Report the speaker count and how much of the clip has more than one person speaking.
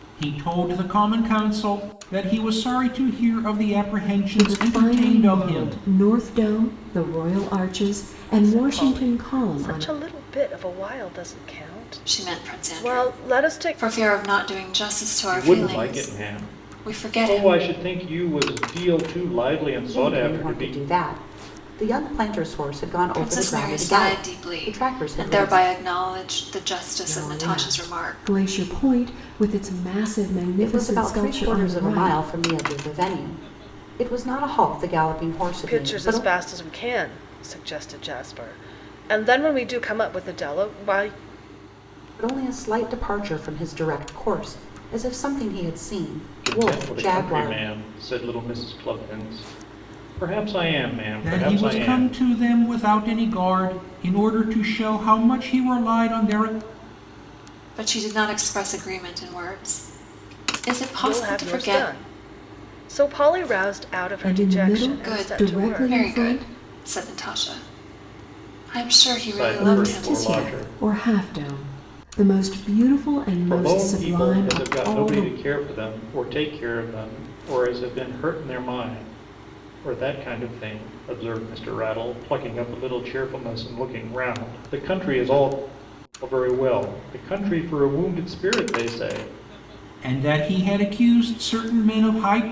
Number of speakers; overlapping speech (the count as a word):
six, about 25%